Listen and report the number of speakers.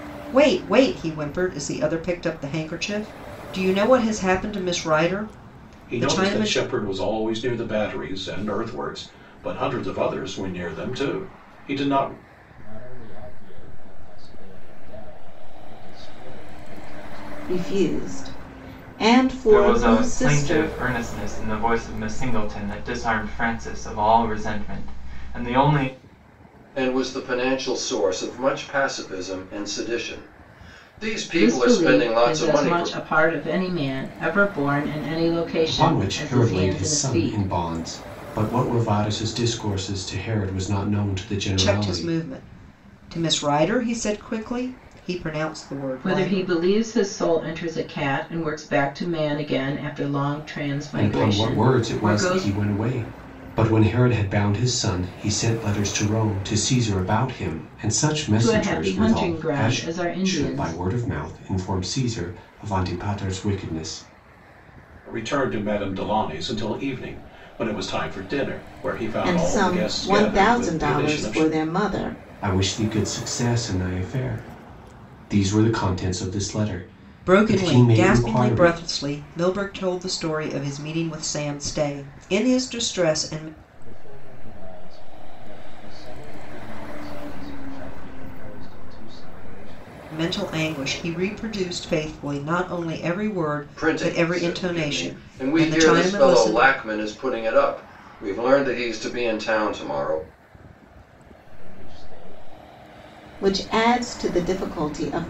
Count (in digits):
8